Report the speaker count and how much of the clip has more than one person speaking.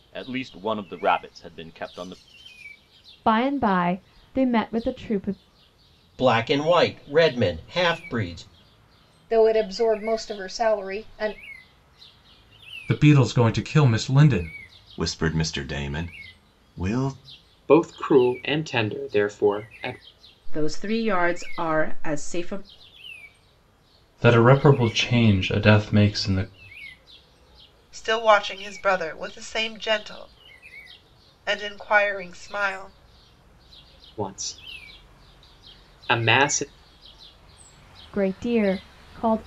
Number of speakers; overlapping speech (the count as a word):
ten, no overlap